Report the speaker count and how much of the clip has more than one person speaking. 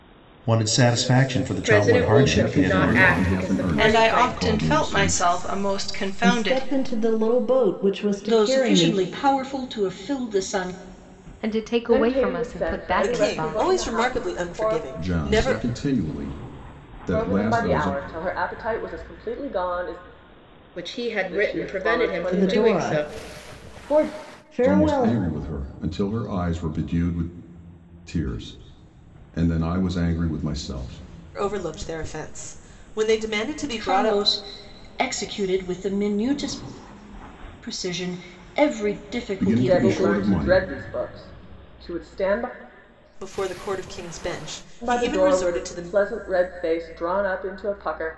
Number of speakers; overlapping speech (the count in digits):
9, about 33%